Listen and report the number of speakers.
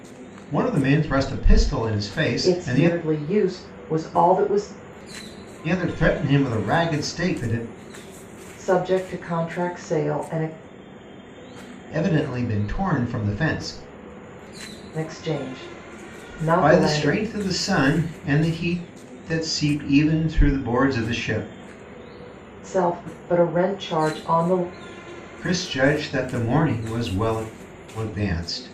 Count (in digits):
2